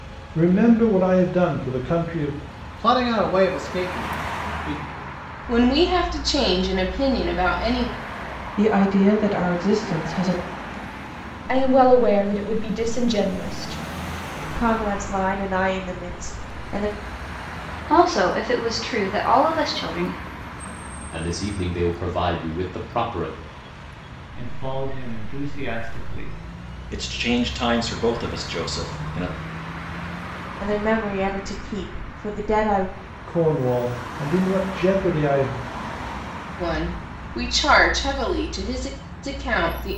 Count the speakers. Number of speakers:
10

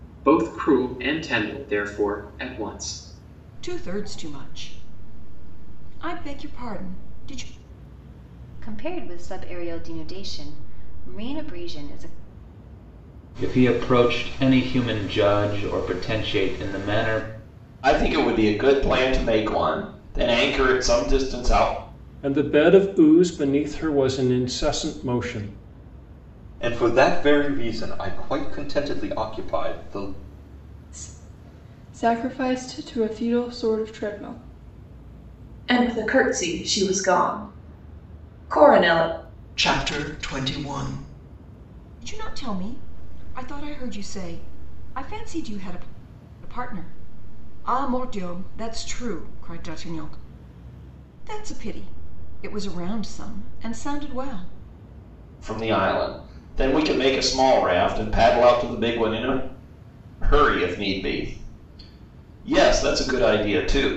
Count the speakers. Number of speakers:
10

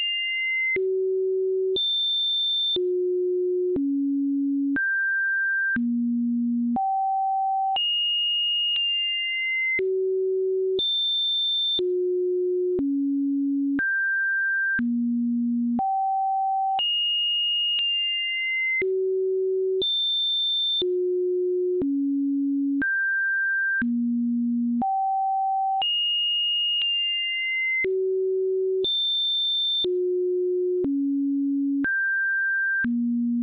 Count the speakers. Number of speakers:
0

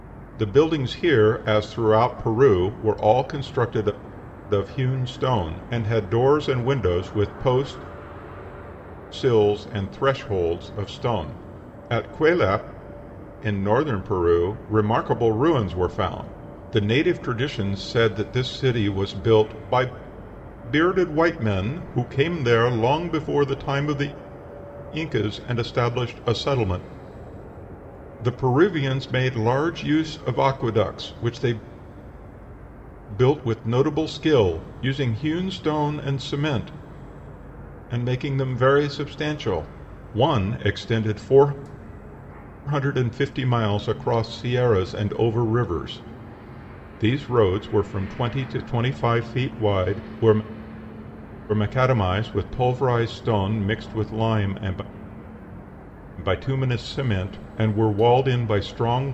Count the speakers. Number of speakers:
1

